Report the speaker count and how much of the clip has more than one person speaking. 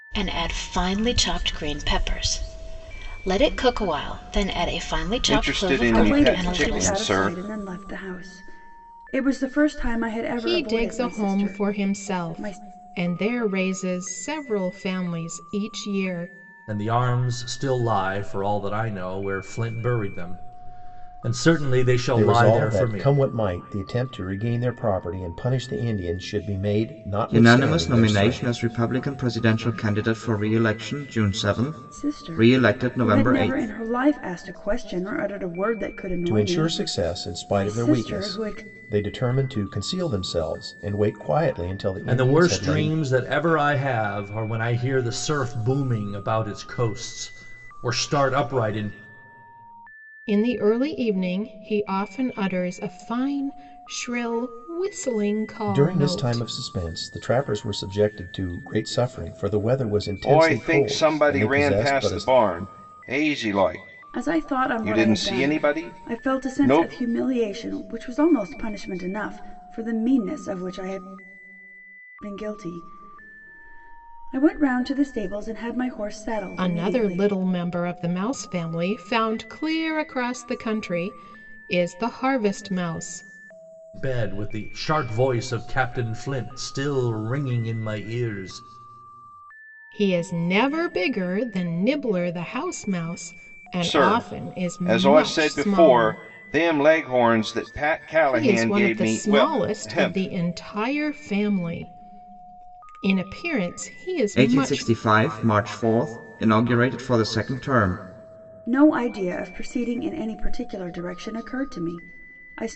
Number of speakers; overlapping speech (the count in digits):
7, about 21%